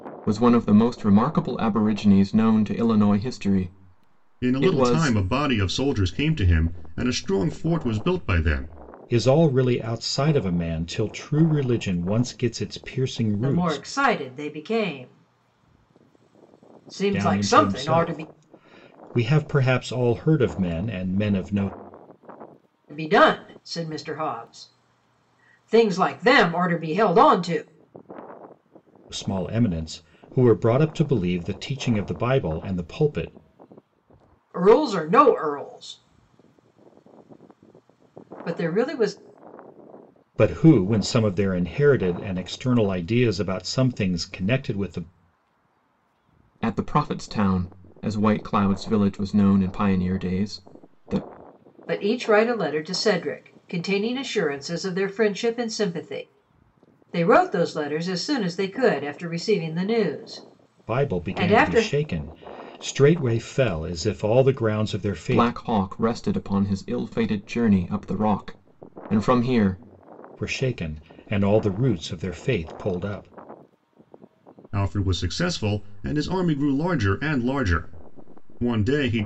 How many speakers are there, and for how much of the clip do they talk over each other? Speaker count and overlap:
4, about 5%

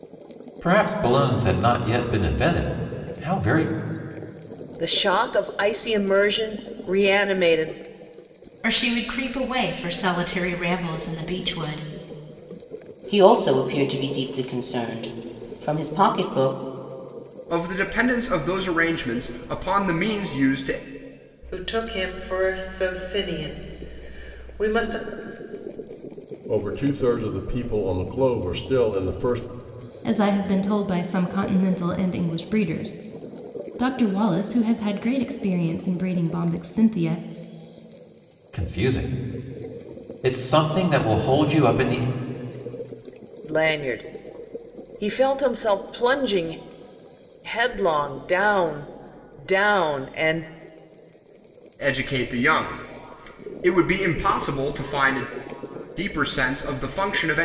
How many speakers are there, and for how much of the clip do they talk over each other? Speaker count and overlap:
8, no overlap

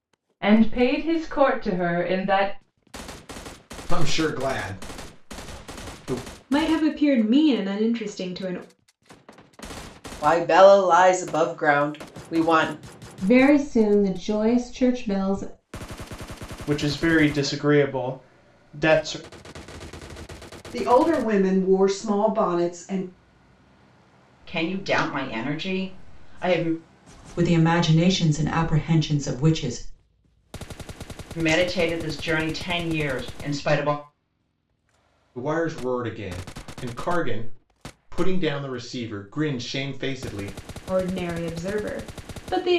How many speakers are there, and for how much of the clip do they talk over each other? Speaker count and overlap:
9, no overlap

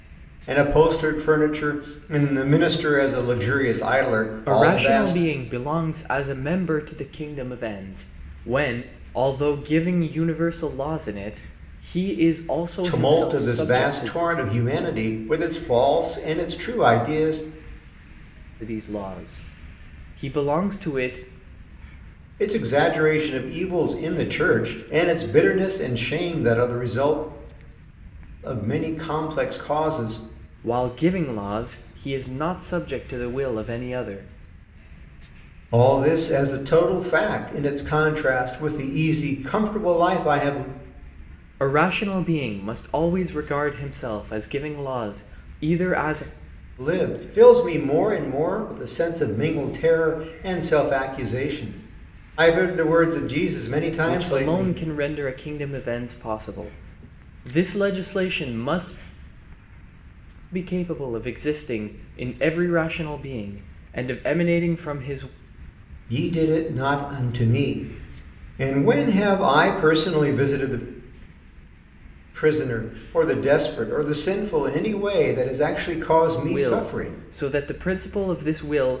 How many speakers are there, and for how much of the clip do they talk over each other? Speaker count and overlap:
2, about 5%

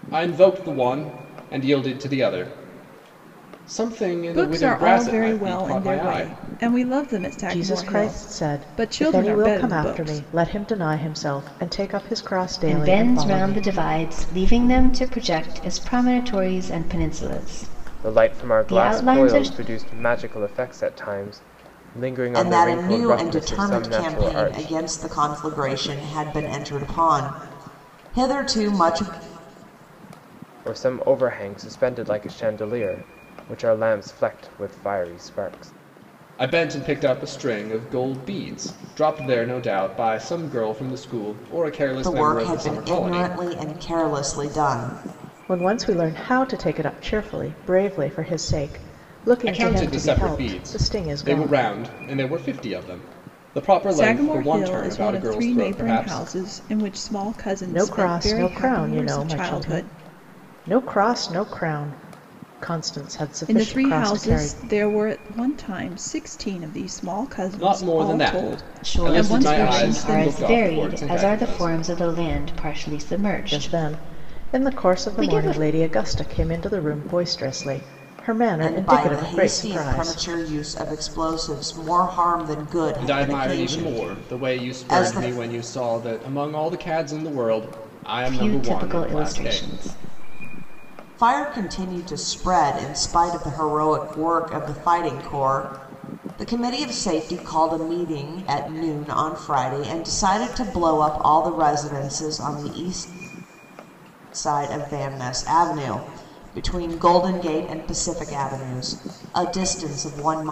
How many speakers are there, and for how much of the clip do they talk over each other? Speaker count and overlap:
6, about 28%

